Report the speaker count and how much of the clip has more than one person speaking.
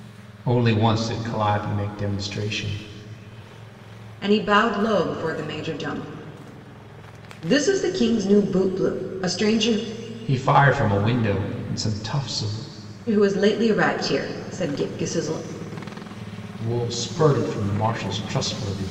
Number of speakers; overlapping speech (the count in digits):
2, no overlap